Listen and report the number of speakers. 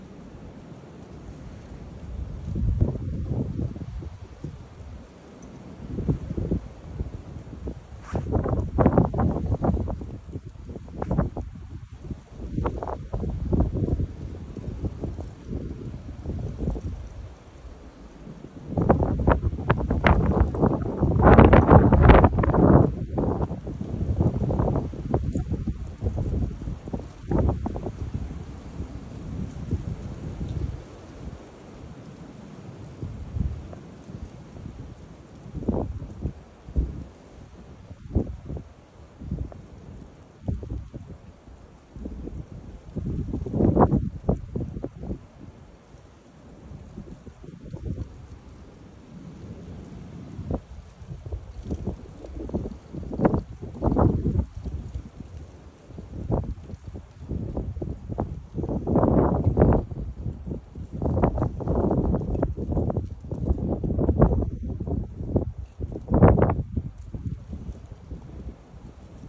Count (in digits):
0